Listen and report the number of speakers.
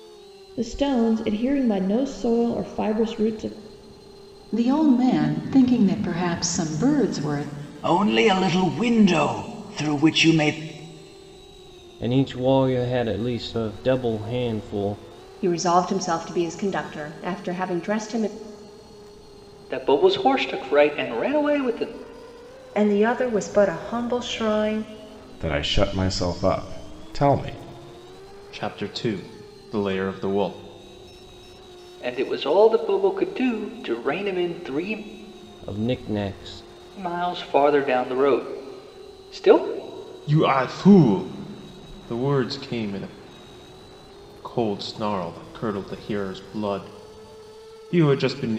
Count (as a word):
nine